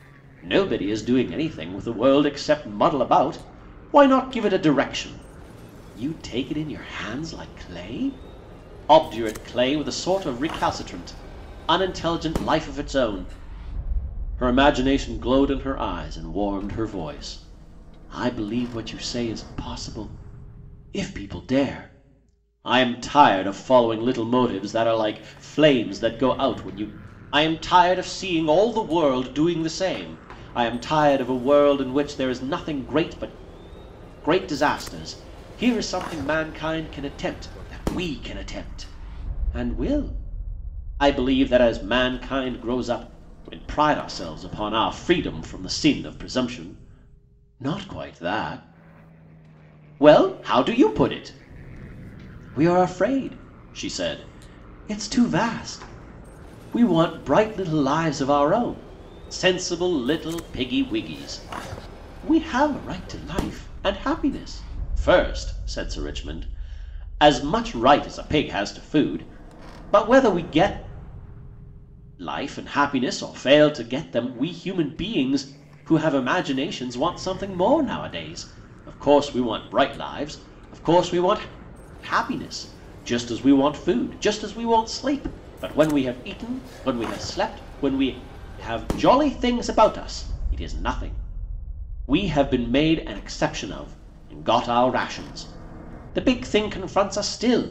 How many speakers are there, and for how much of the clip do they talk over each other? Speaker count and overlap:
one, no overlap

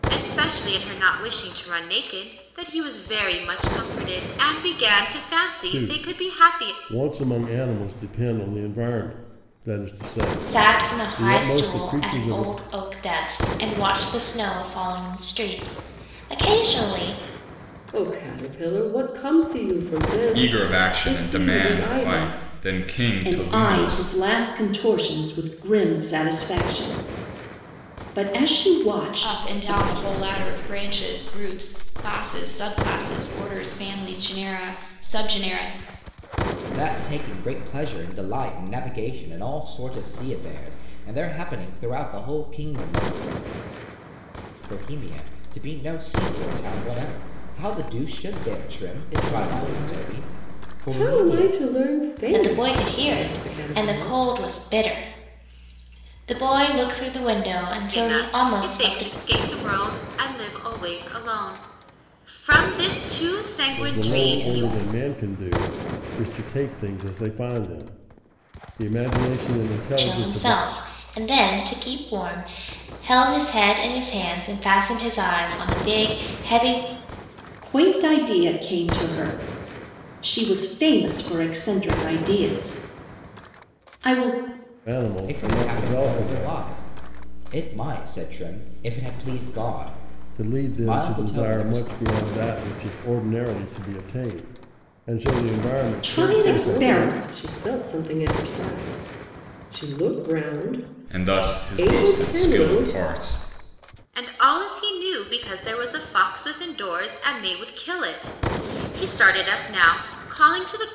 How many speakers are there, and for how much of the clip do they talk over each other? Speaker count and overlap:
eight, about 18%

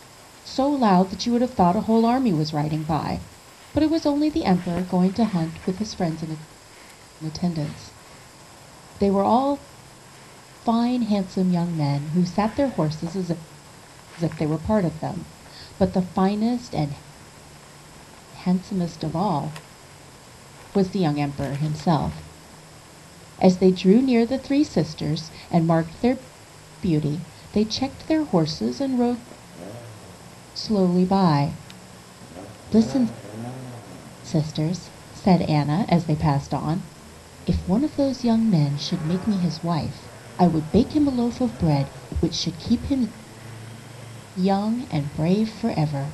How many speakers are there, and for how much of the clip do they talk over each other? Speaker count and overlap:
one, no overlap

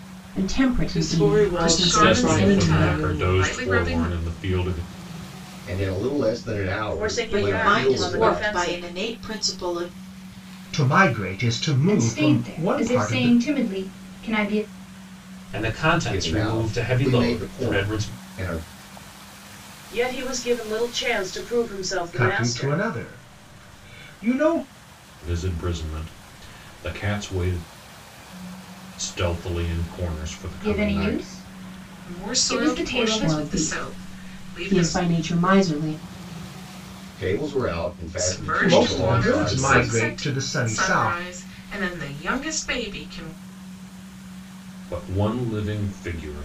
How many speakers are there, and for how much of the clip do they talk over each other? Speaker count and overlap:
ten, about 35%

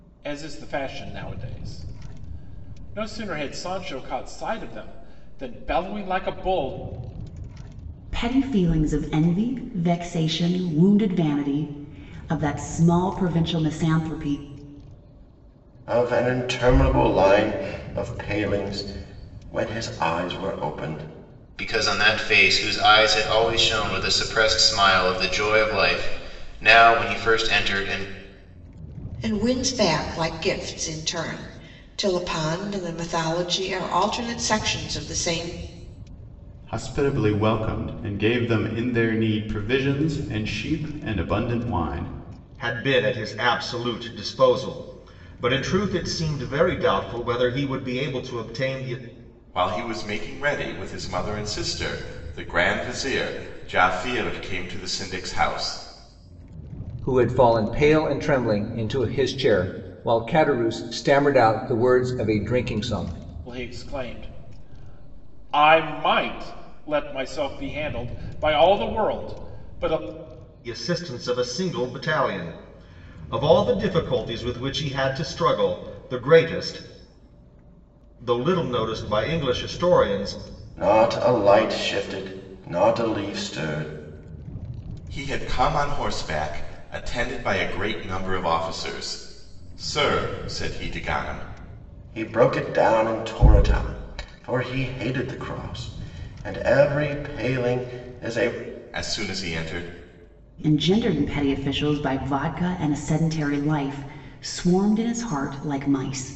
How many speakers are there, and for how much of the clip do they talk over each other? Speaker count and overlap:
nine, no overlap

